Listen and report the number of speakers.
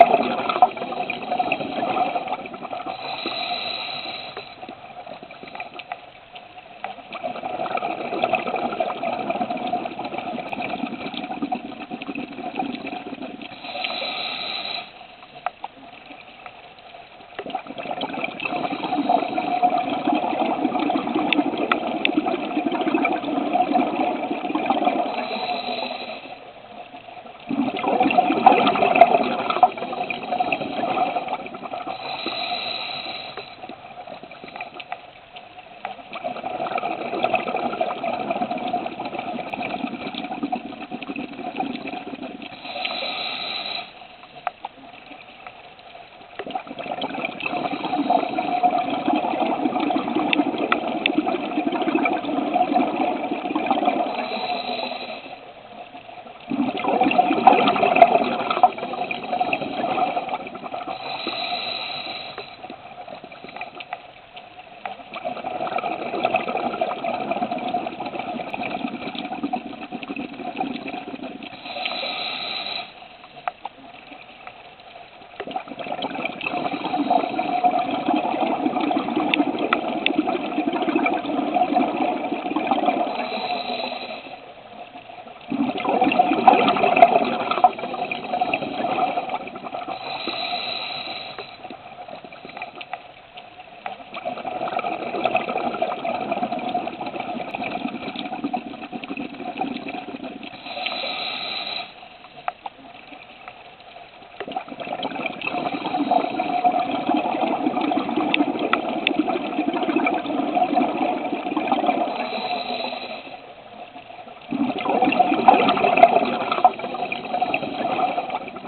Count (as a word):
zero